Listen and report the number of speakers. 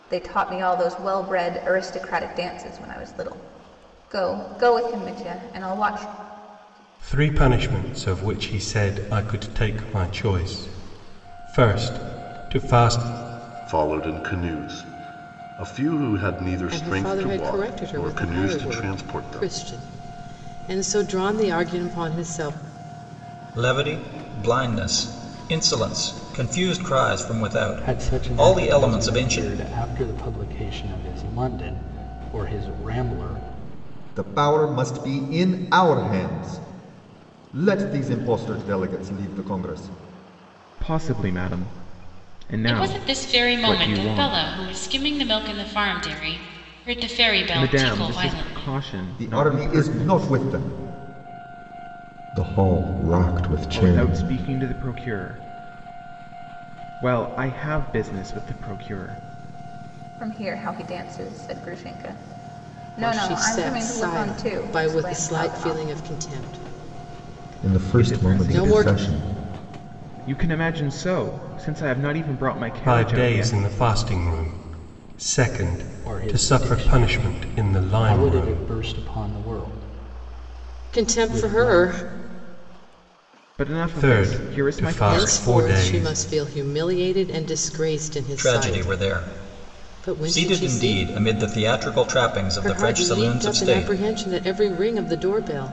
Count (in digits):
9